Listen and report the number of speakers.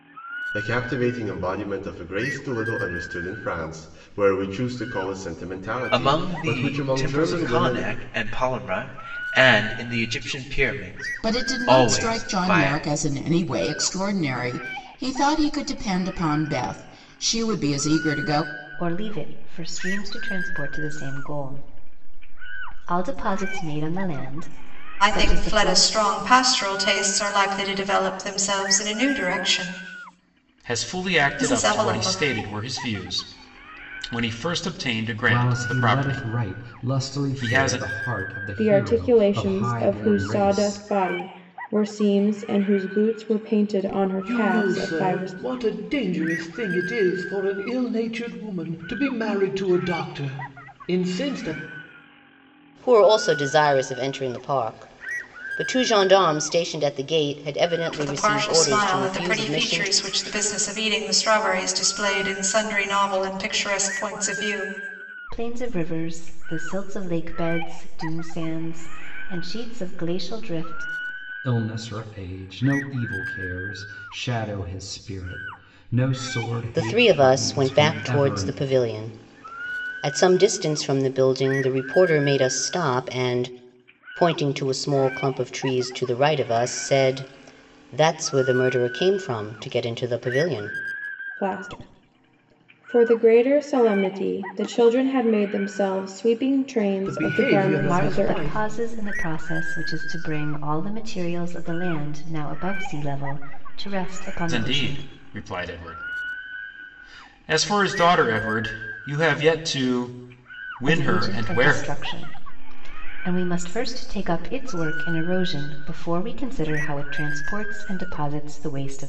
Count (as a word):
ten